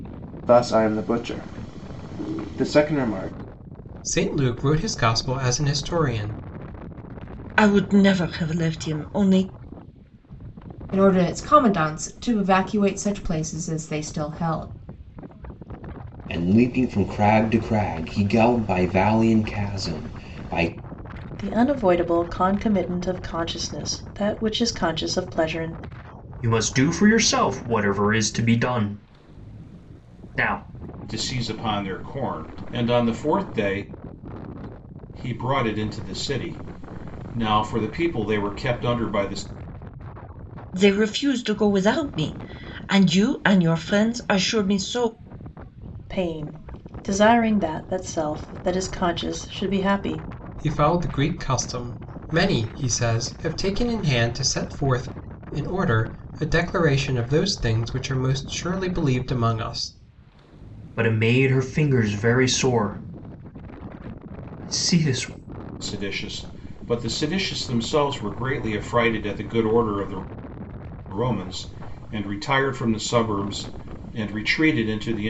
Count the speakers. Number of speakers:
8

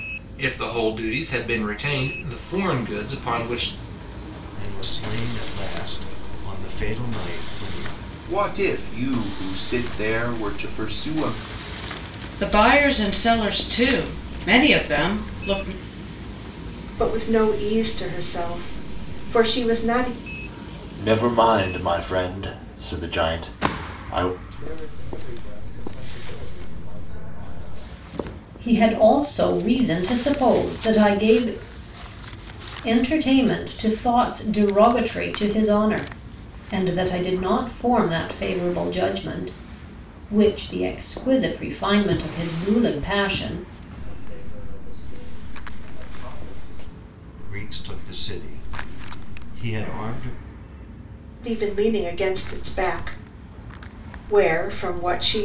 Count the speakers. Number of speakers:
8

